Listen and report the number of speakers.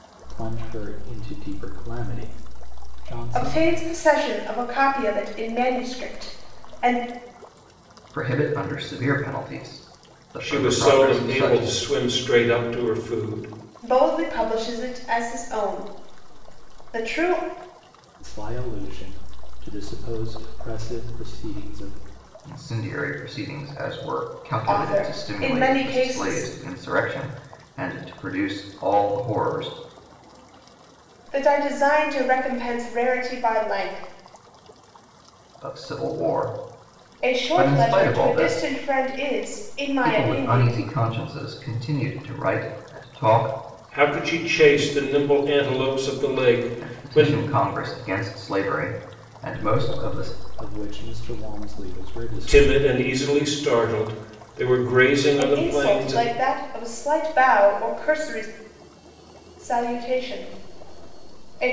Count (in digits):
4